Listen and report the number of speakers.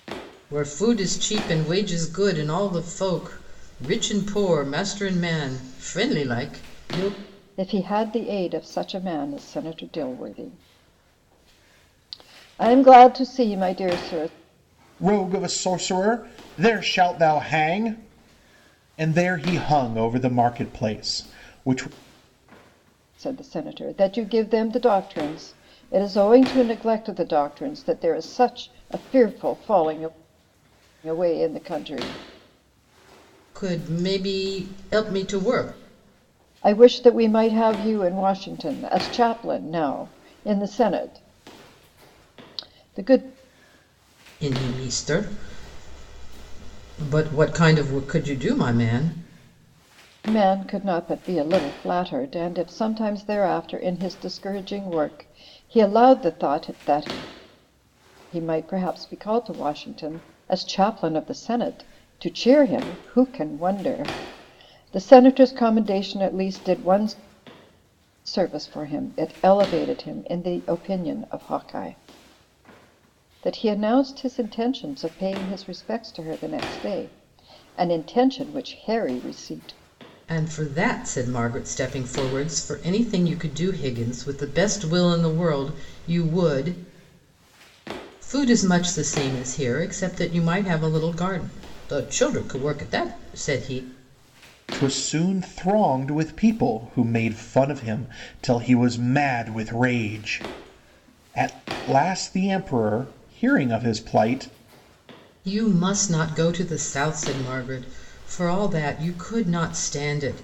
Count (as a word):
three